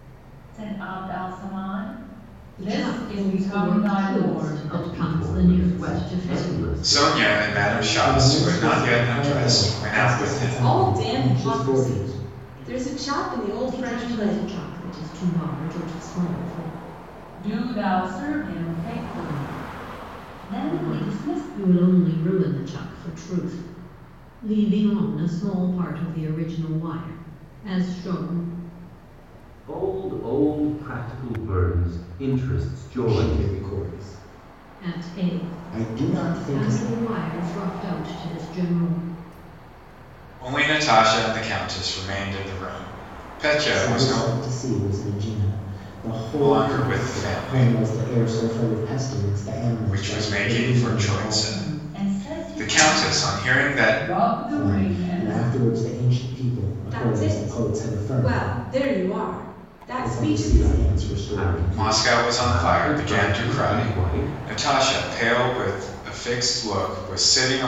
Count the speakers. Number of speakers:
6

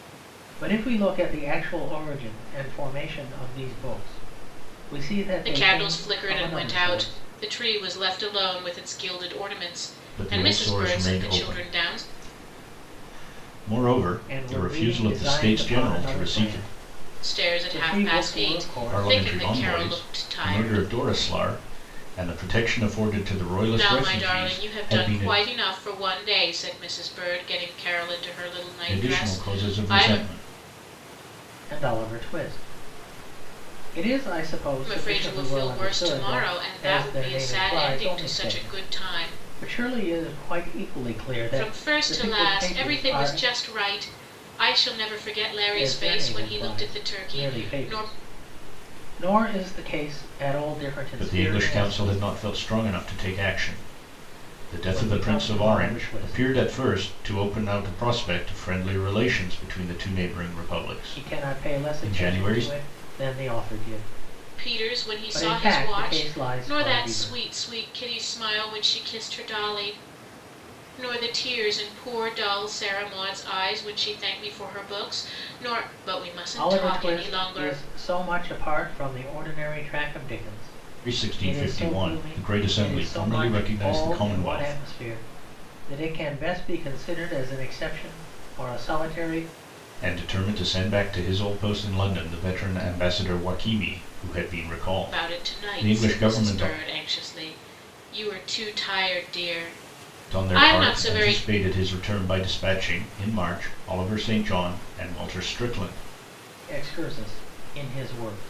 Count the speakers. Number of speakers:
3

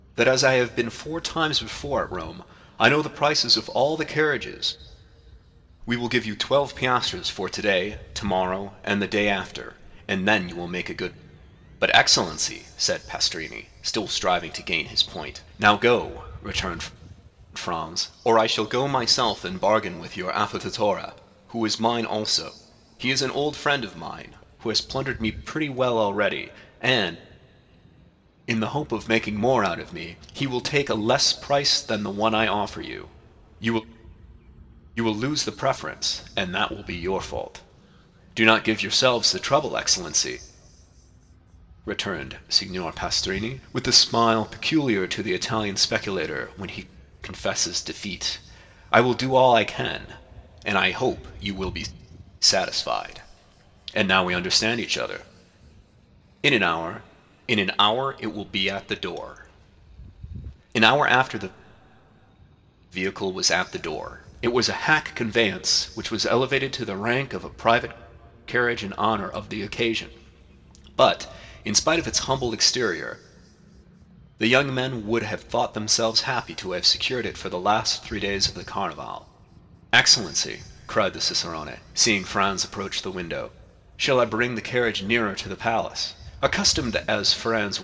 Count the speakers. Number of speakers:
1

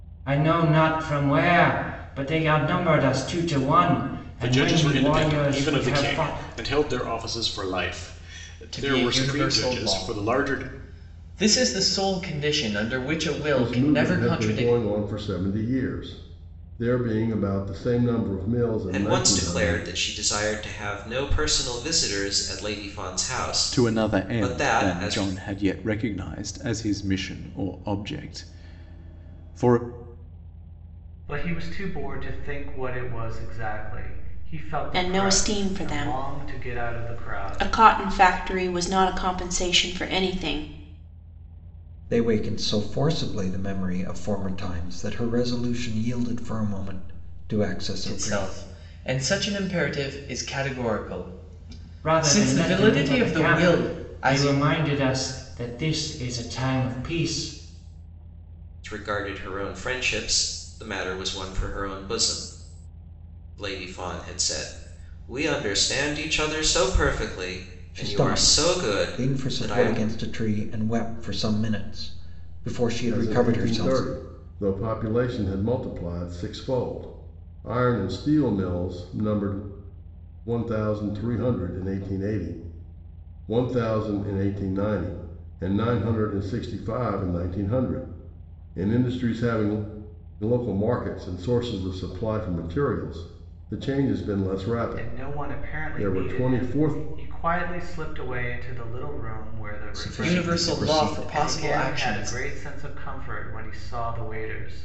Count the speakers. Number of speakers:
9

